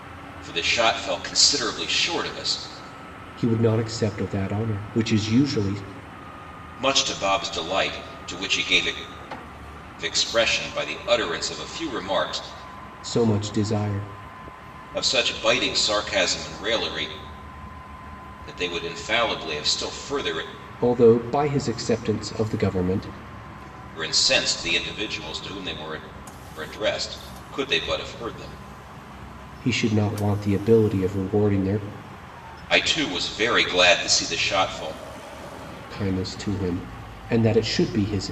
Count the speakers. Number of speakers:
two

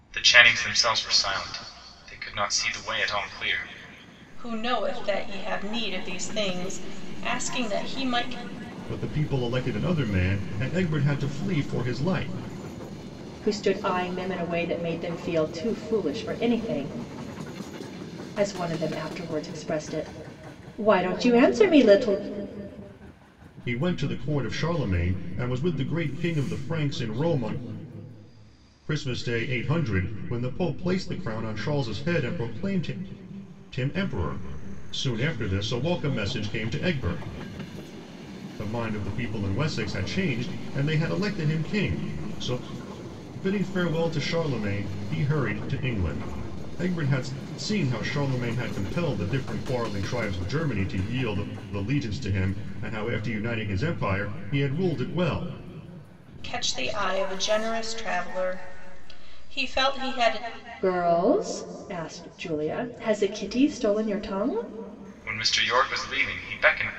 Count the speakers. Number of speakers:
four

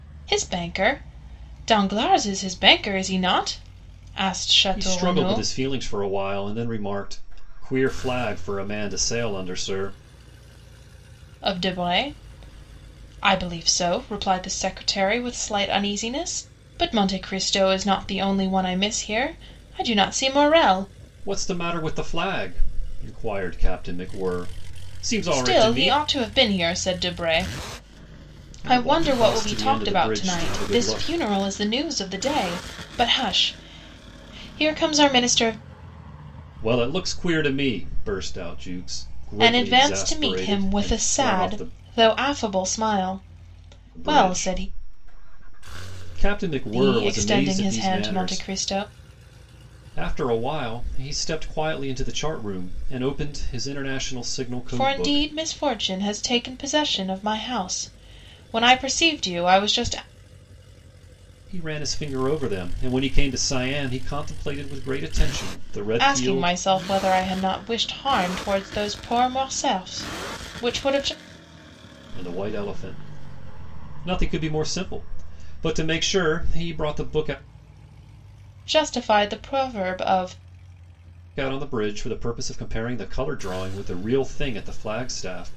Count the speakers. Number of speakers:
two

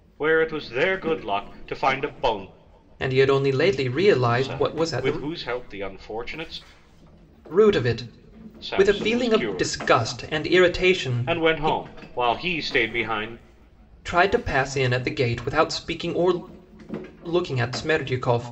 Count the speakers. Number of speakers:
two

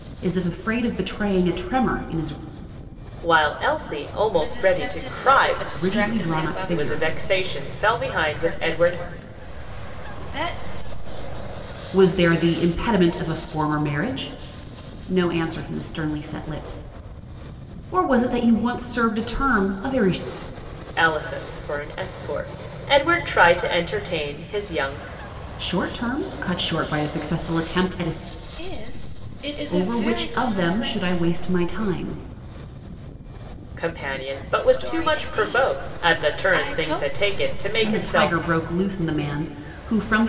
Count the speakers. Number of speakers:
three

